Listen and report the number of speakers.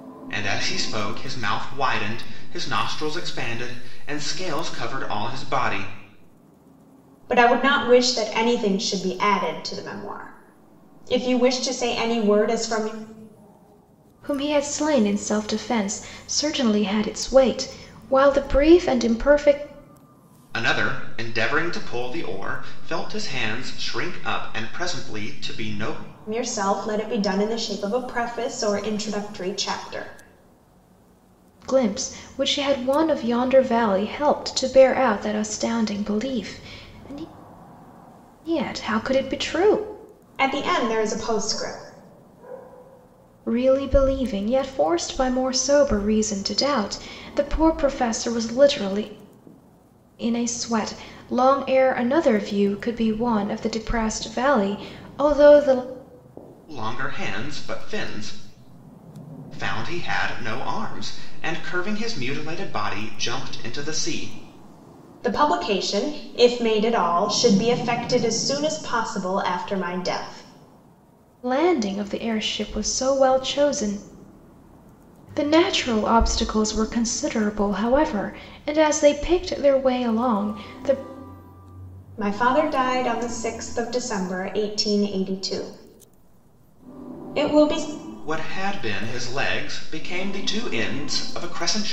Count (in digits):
3